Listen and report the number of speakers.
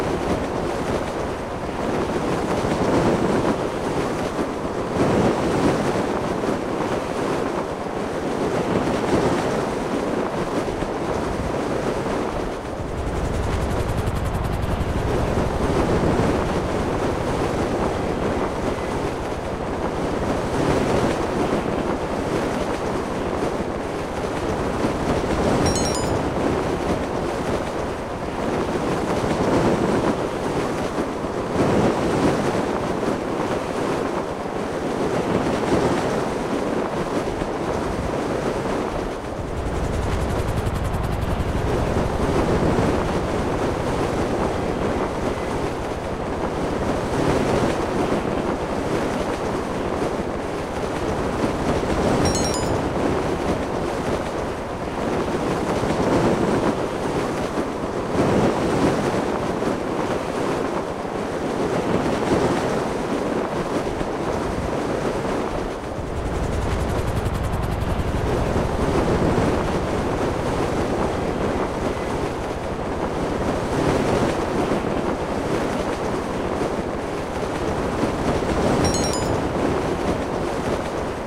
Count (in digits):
0